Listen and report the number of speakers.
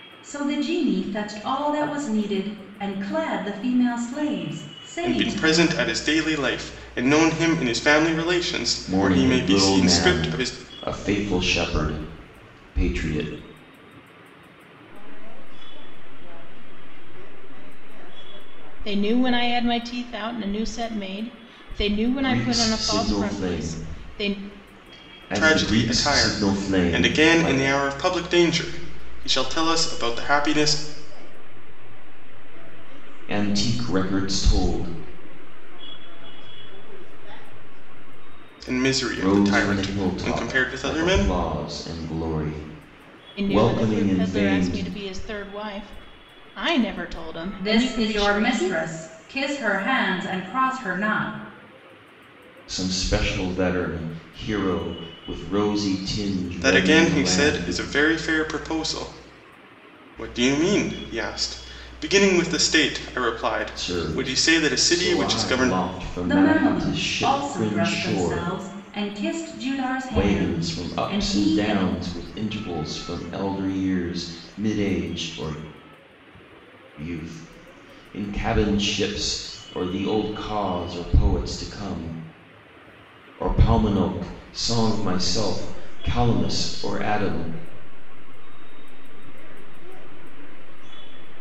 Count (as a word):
five